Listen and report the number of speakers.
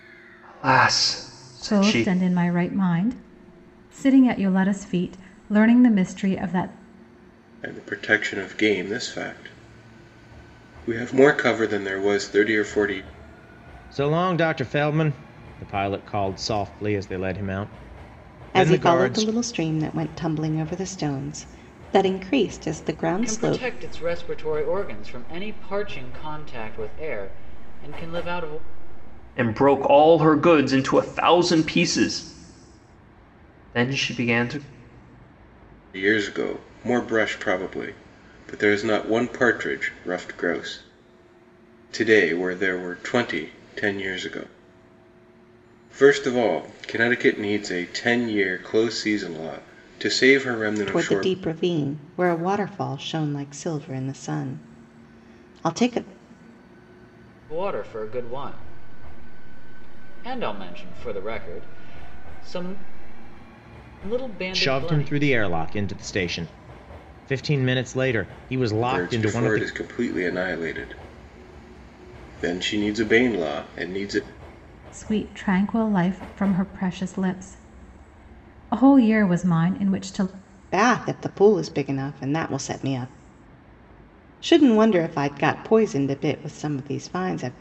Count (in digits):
6